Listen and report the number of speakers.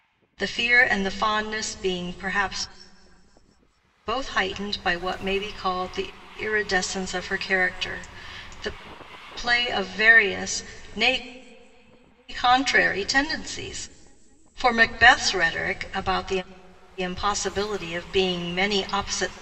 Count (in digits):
1